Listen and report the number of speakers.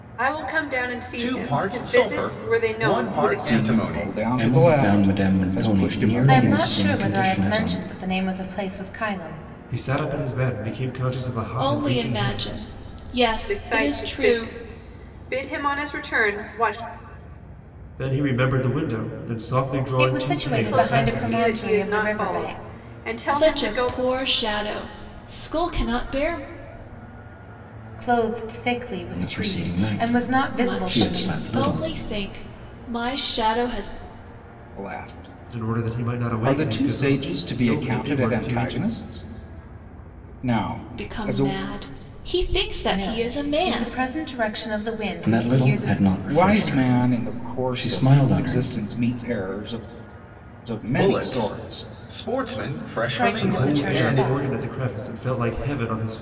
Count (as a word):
seven